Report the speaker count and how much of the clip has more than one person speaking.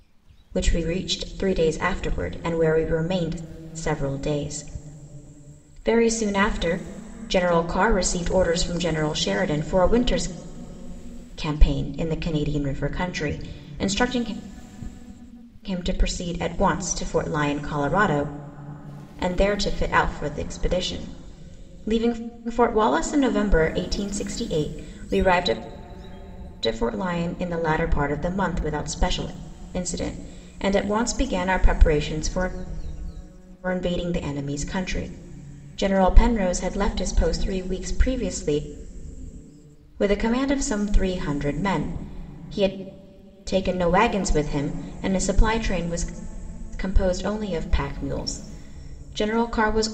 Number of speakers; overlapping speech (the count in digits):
1, no overlap